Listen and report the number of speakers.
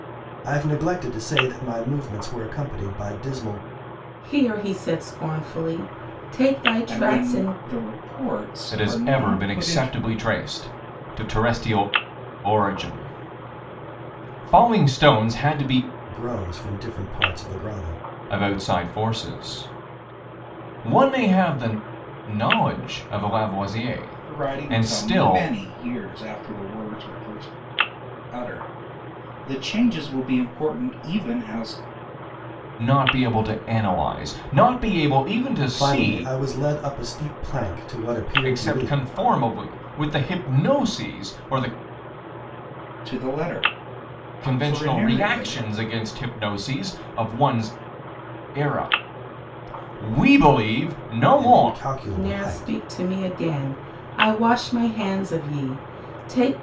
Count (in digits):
4